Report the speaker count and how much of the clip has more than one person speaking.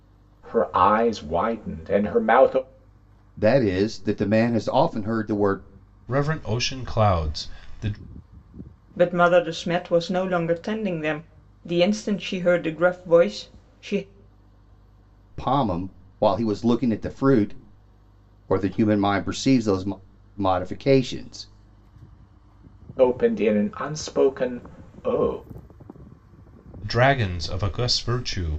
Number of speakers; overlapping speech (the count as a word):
four, no overlap